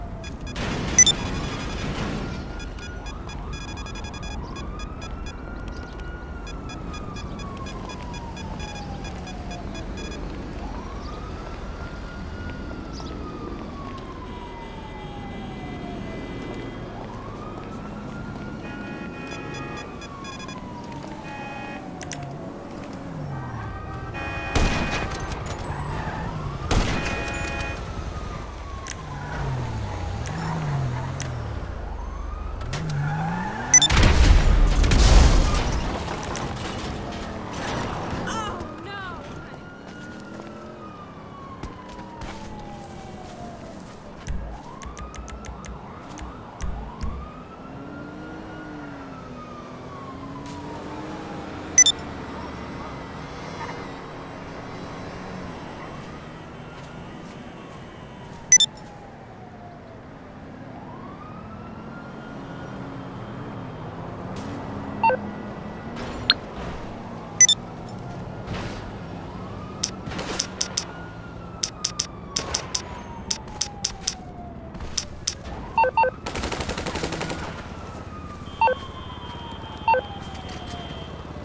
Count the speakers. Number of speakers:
0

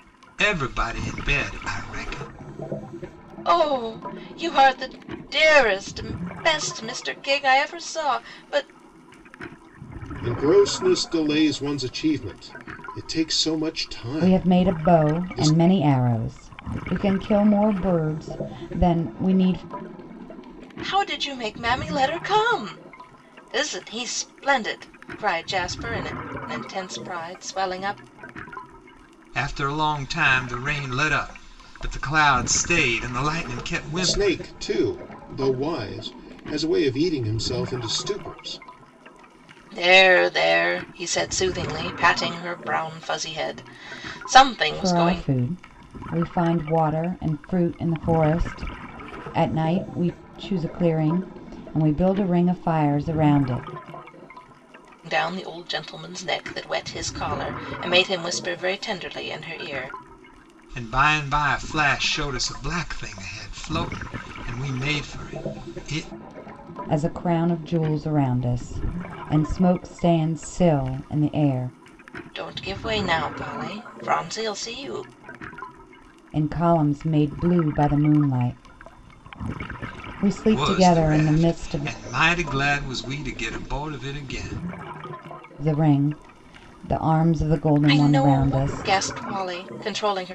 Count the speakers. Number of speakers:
4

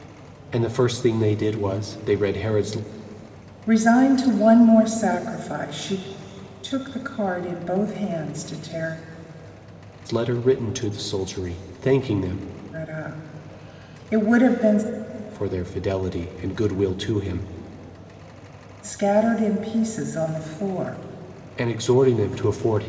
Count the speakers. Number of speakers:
2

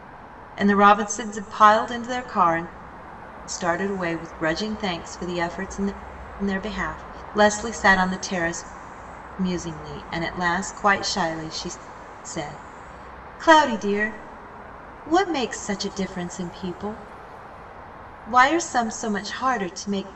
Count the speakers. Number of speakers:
1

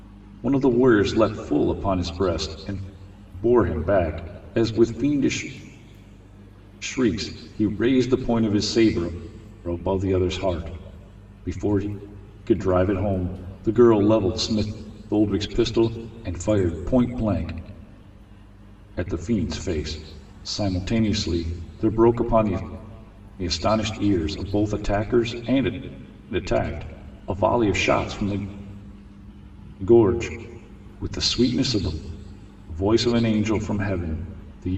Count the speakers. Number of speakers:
1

